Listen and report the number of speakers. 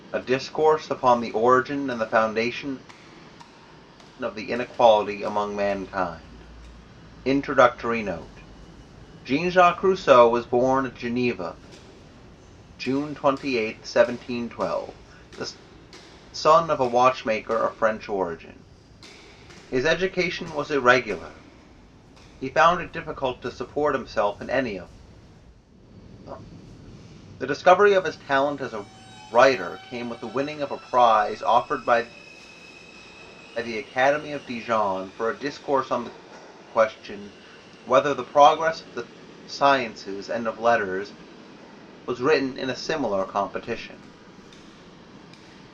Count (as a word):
one